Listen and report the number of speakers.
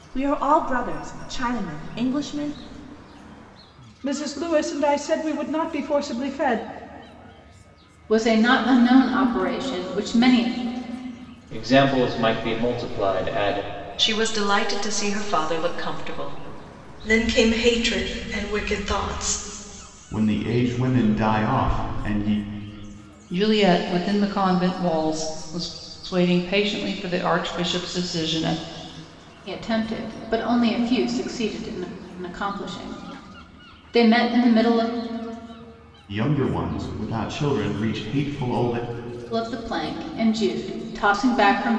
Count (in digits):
8